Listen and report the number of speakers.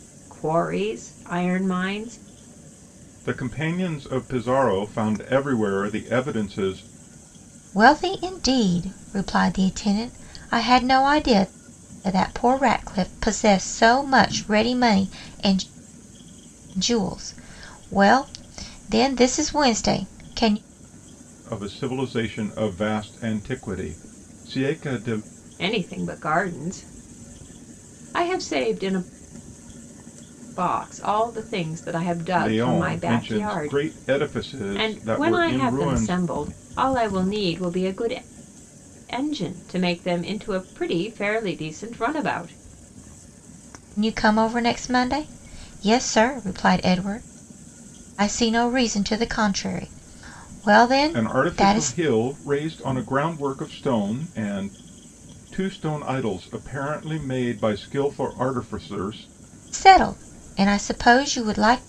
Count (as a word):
three